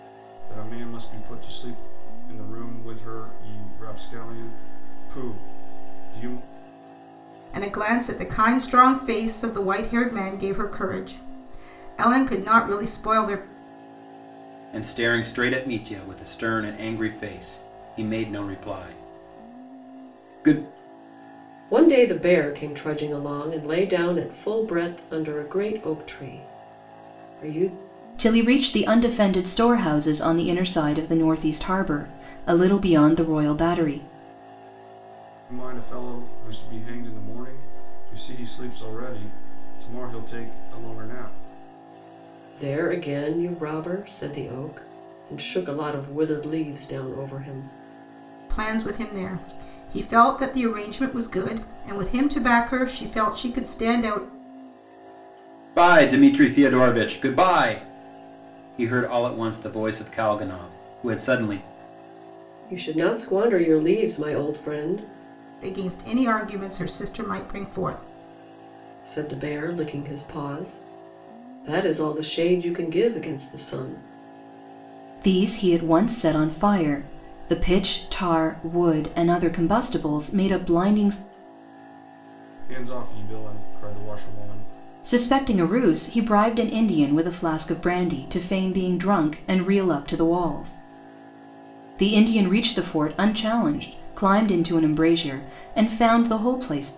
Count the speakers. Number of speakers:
5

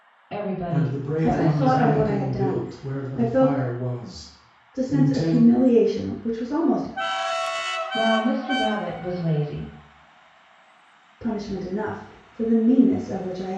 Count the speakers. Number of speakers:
3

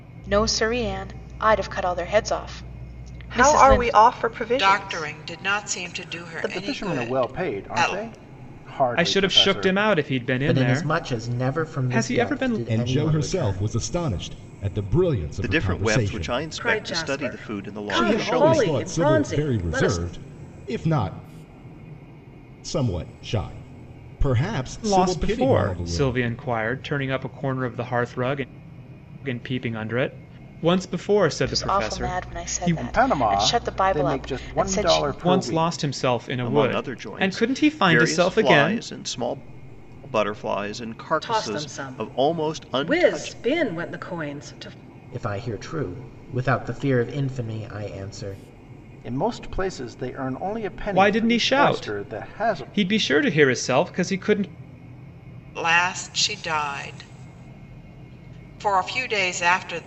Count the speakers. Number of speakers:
9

